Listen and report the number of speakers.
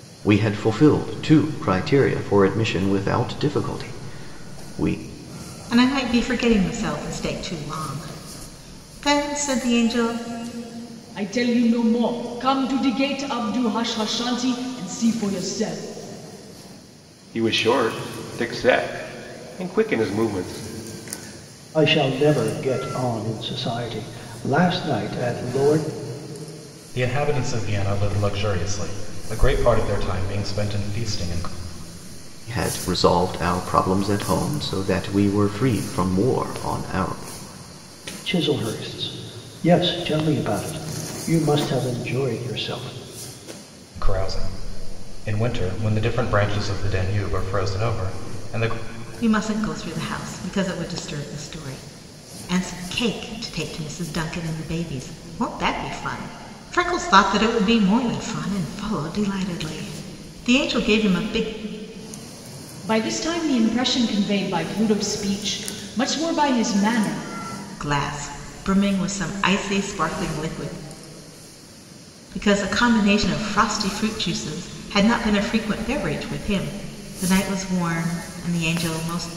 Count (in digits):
6